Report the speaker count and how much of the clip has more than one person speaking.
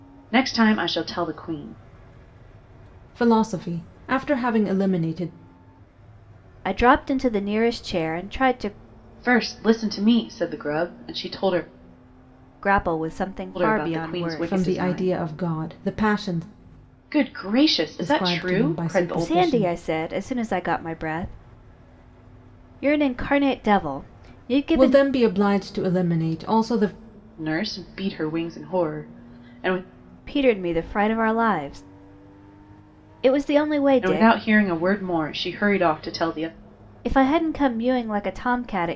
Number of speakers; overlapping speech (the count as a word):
three, about 10%